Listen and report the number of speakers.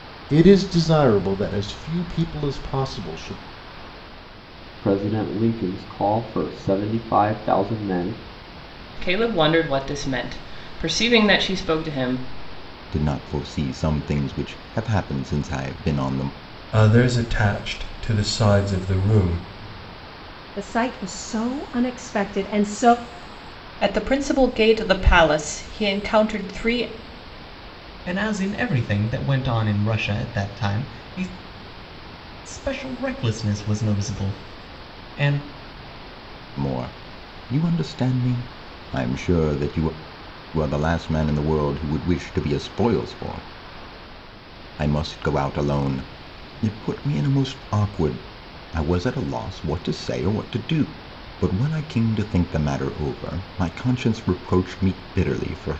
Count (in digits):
8